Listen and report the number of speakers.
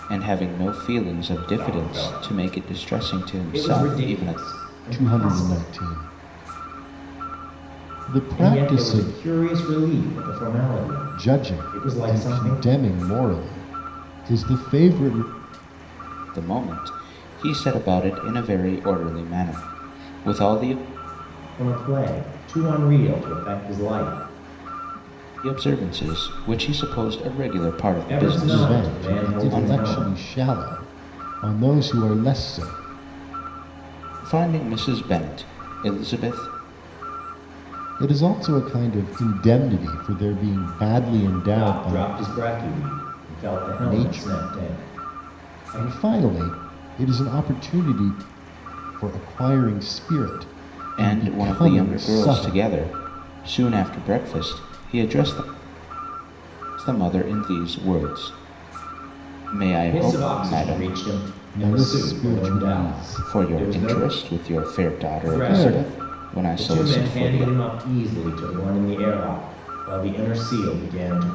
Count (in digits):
3